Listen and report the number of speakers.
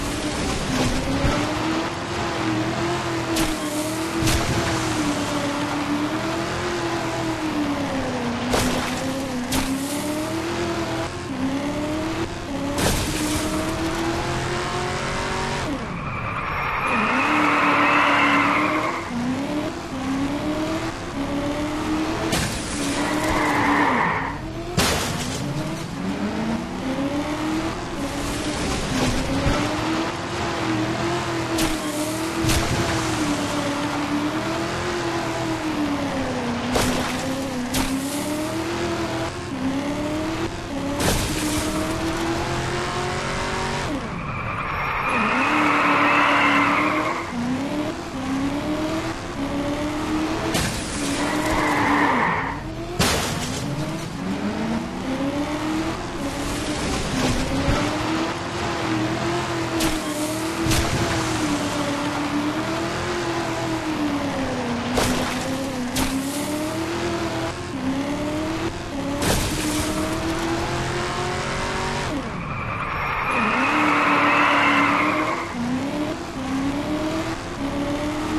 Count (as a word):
zero